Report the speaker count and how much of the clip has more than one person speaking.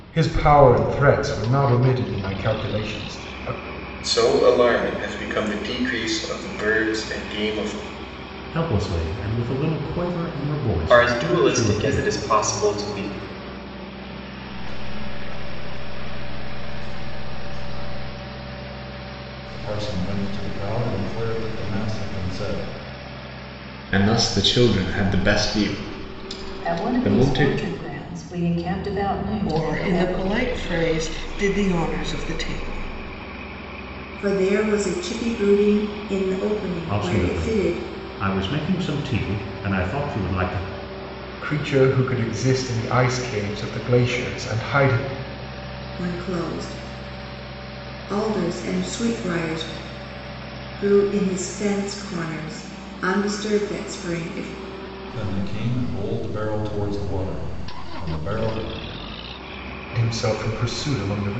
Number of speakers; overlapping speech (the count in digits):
10, about 7%